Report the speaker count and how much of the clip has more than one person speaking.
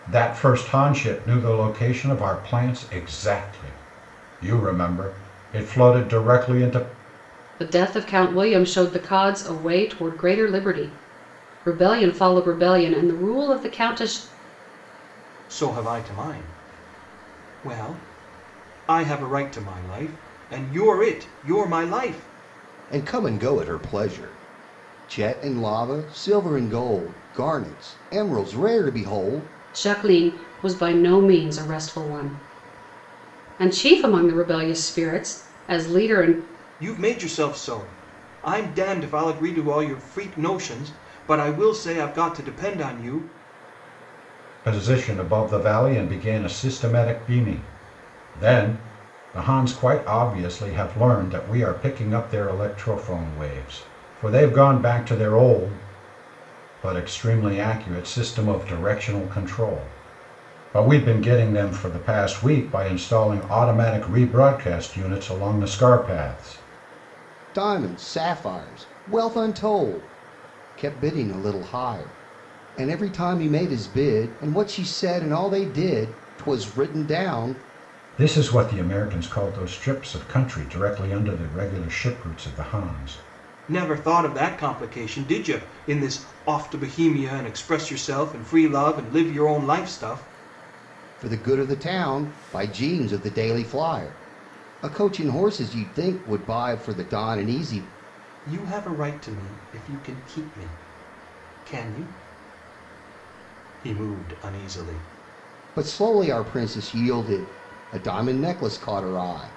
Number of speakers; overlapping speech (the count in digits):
4, no overlap